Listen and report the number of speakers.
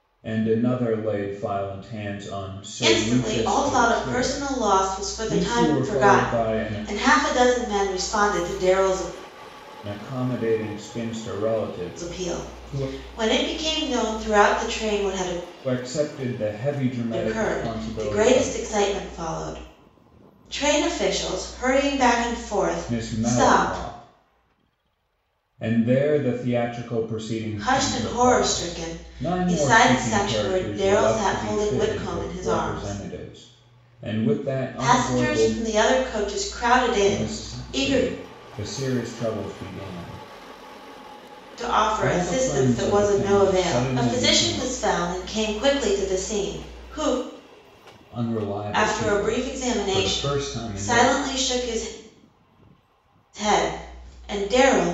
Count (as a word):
two